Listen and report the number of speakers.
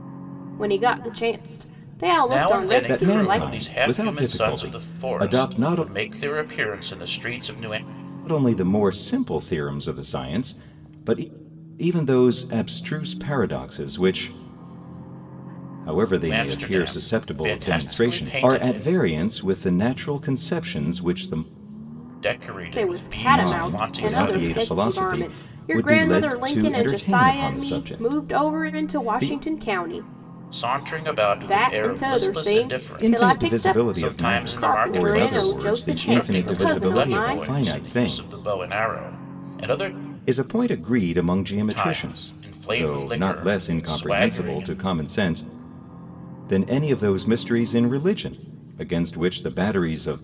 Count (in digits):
3